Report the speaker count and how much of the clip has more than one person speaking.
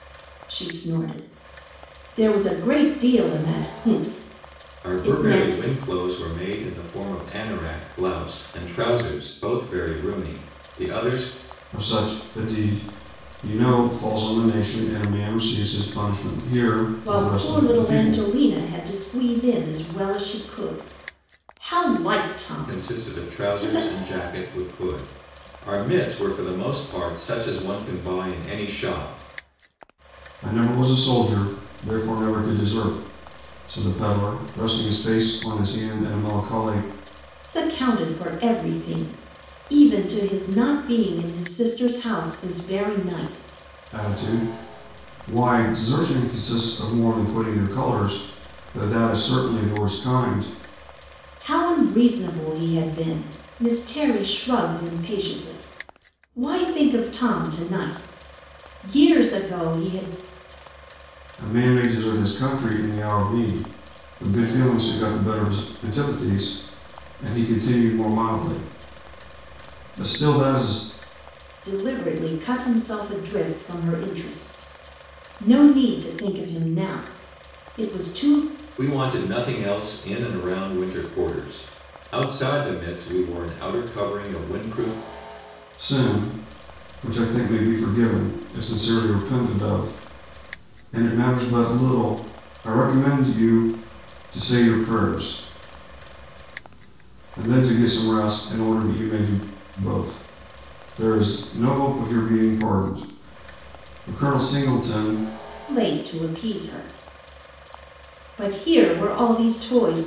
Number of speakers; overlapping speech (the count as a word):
three, about 3%